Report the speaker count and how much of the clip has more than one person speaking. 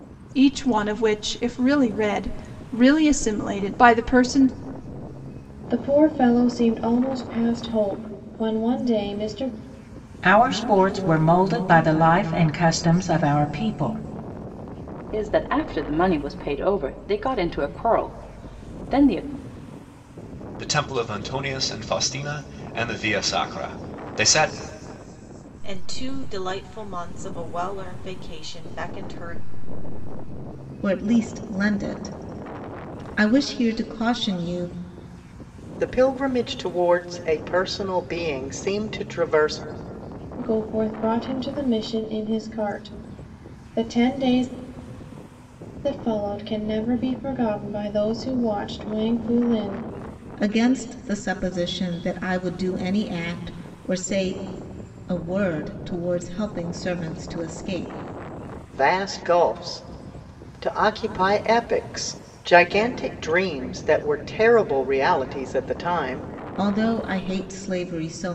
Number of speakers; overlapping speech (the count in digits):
8, no overlap